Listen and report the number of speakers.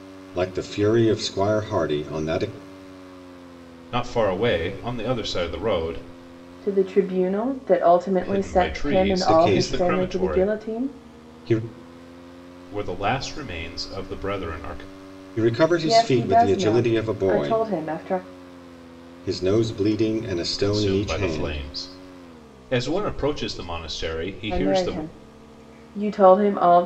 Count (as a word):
three